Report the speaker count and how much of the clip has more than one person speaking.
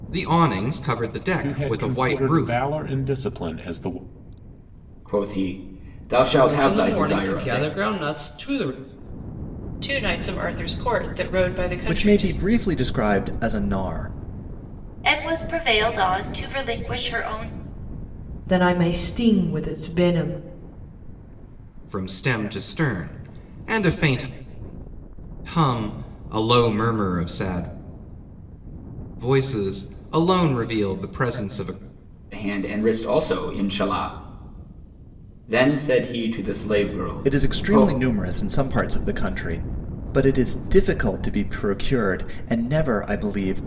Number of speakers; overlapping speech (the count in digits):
8, about 9%